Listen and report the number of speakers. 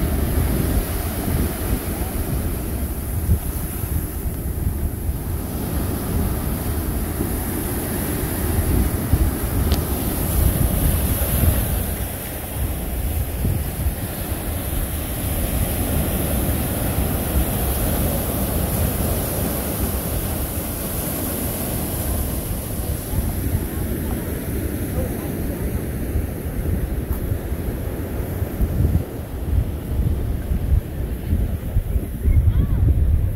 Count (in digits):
0